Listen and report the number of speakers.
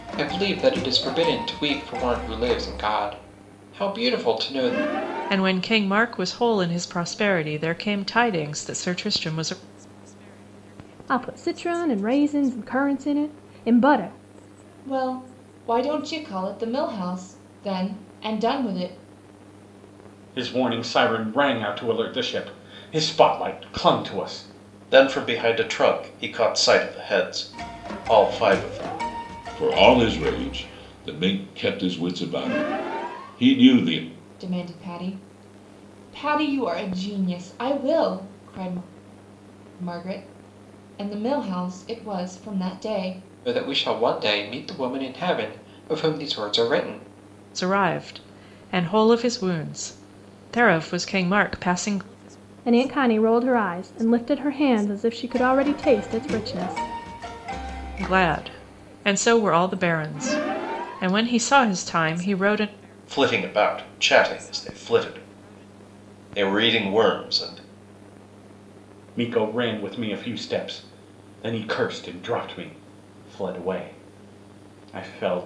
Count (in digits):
7